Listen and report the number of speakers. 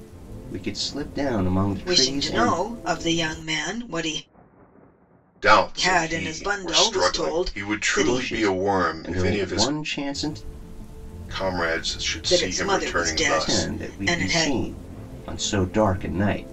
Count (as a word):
three